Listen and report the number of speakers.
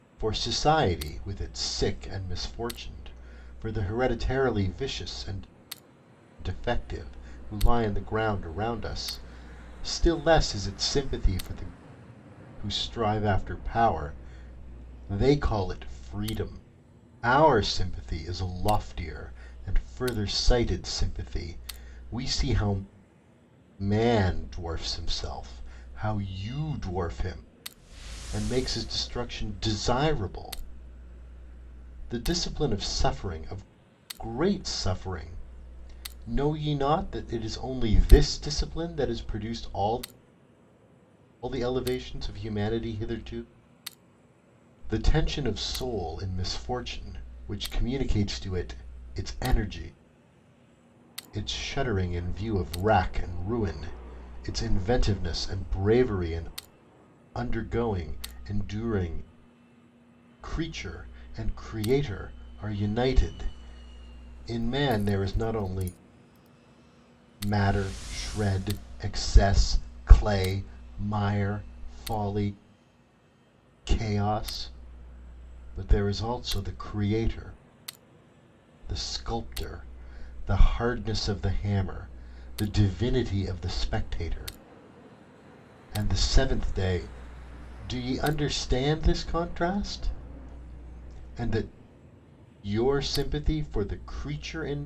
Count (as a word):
one